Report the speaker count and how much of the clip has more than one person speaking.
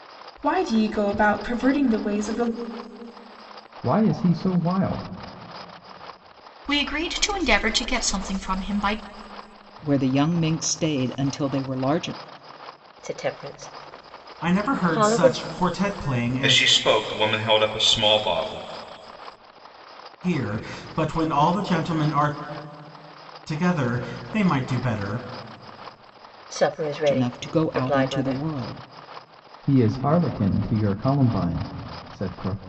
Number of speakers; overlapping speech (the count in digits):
7, about 8%